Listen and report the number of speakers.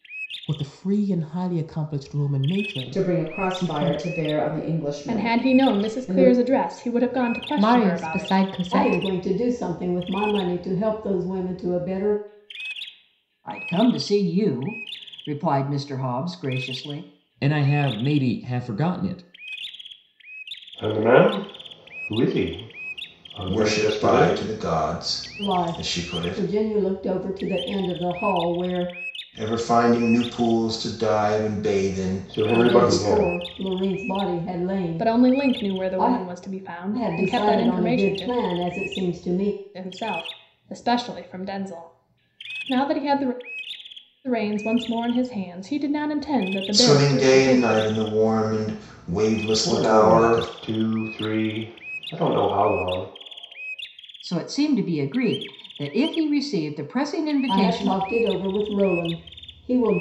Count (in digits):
9